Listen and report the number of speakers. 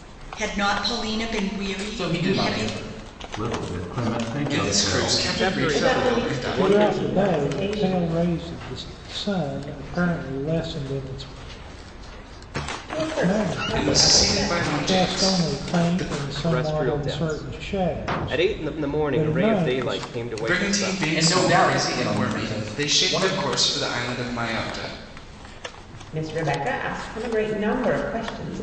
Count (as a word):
seven